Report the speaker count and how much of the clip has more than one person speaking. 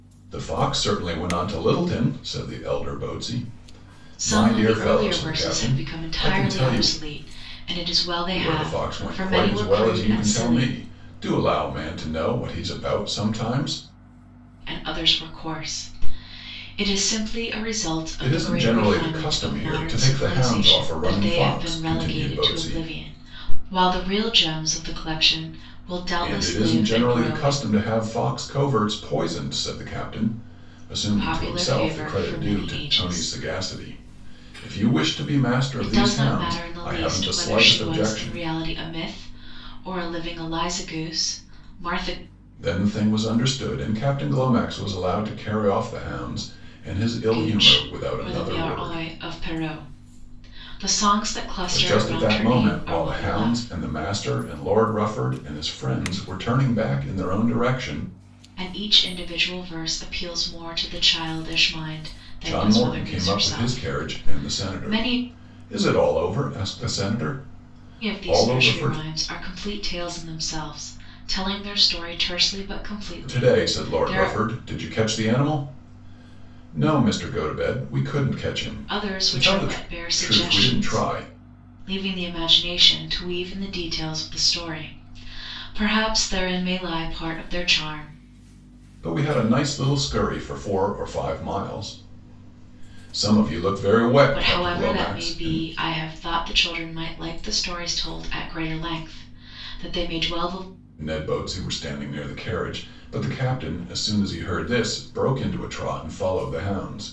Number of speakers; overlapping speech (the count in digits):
2, about 26%